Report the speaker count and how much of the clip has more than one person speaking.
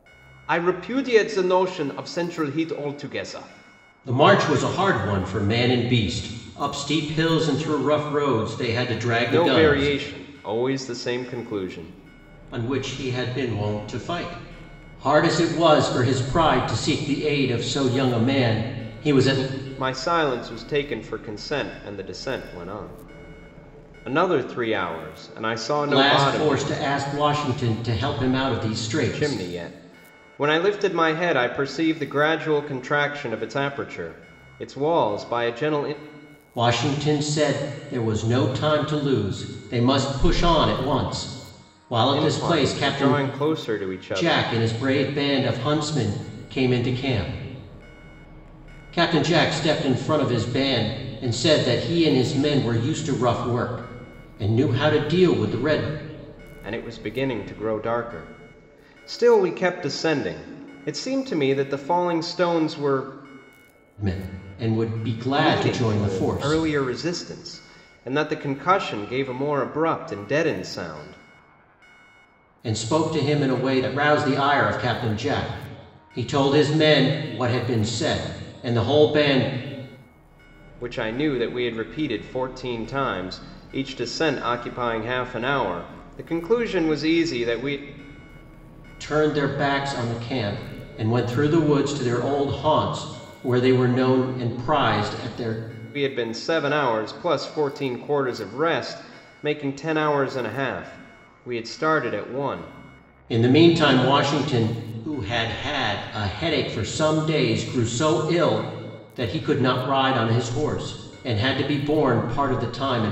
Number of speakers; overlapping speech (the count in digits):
2, about 4%